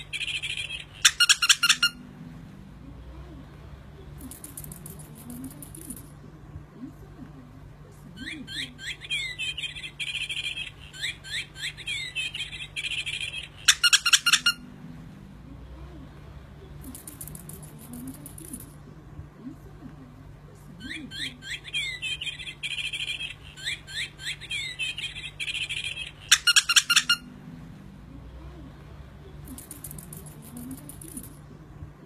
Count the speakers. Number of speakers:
0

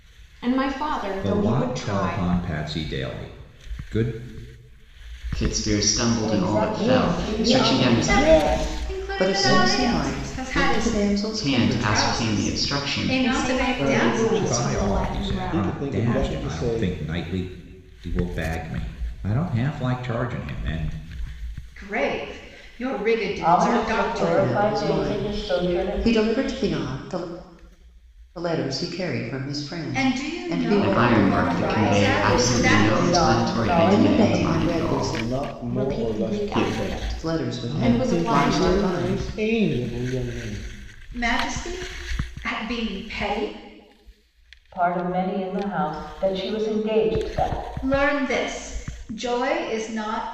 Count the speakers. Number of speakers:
7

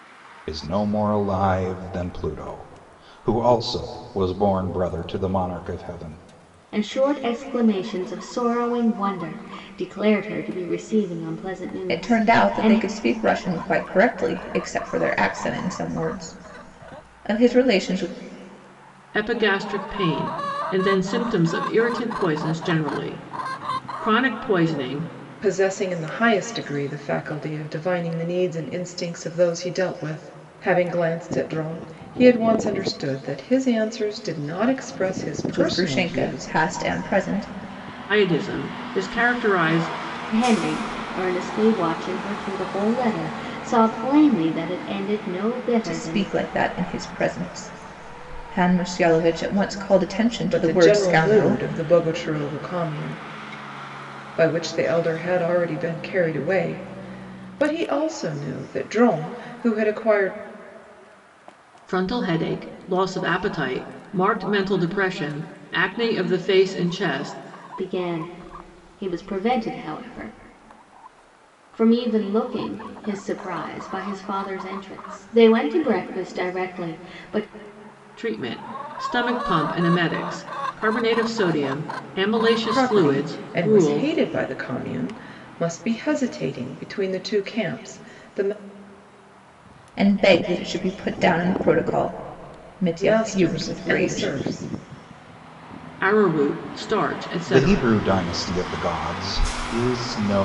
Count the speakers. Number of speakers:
5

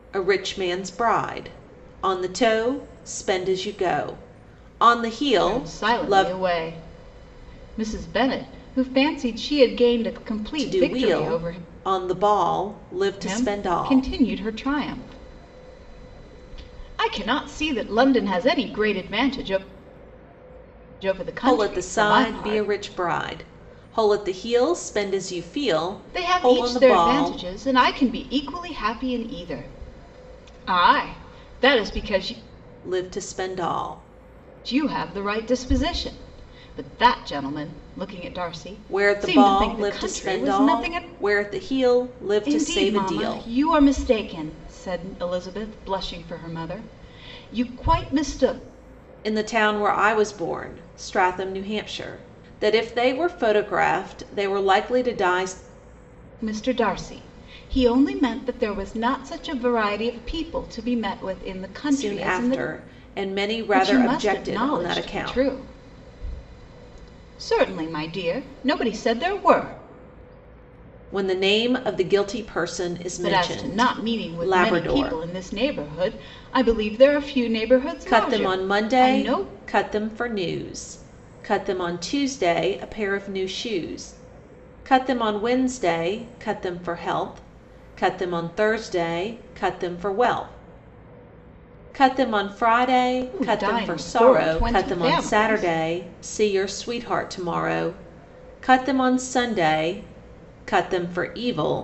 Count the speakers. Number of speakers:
2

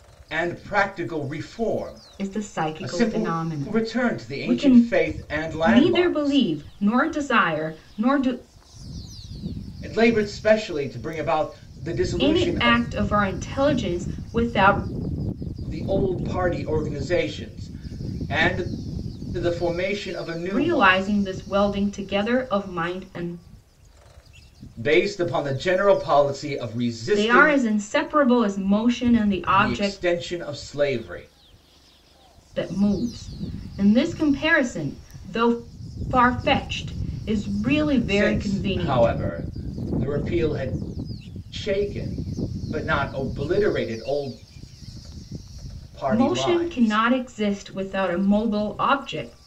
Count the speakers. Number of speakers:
2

